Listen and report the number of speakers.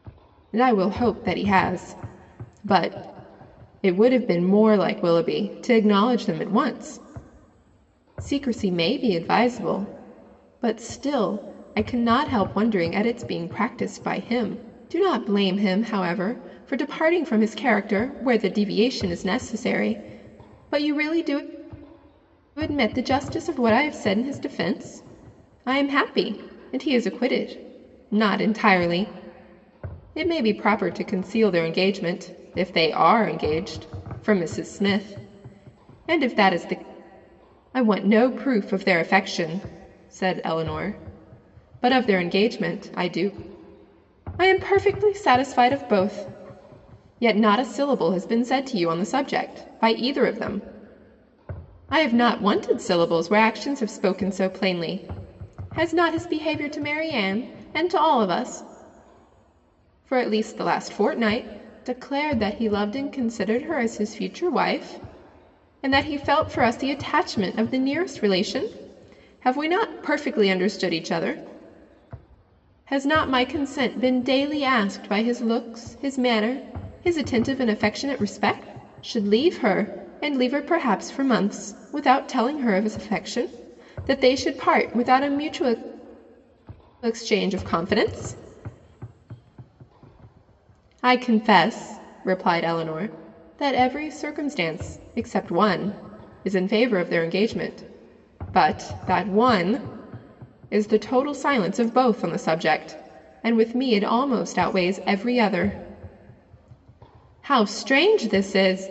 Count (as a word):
one